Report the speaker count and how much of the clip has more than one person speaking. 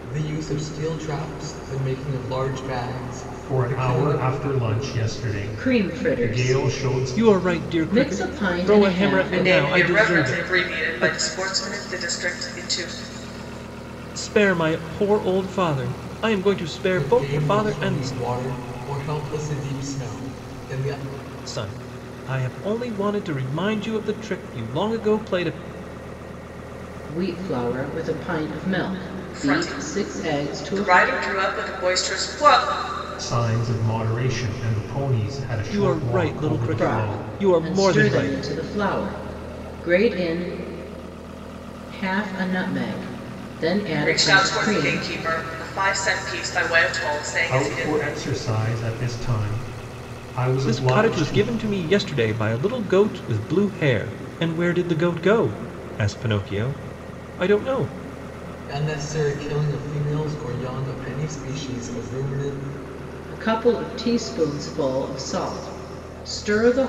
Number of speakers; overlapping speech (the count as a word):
five, about 22%